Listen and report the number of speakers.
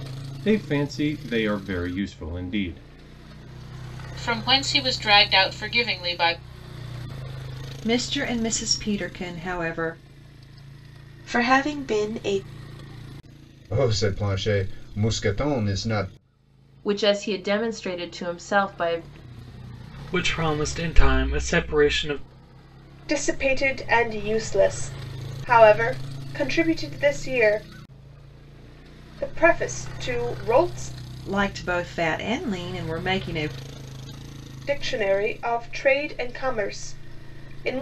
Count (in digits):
8